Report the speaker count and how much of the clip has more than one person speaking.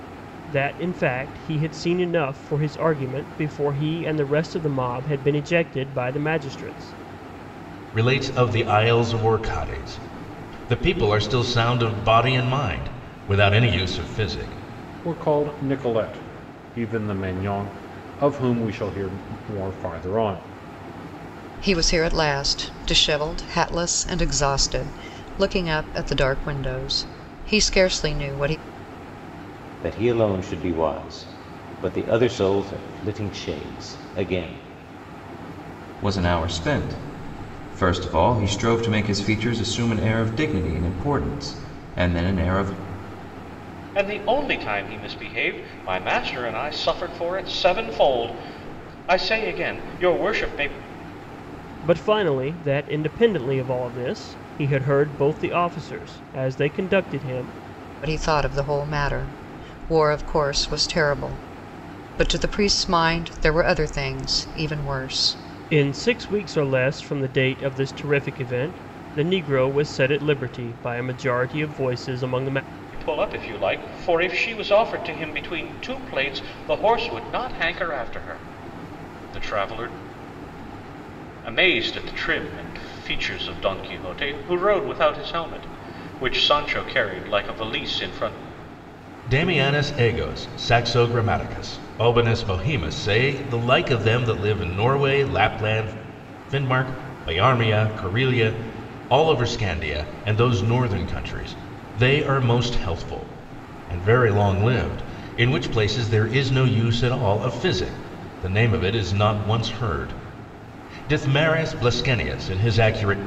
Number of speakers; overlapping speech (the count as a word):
seven, no overlap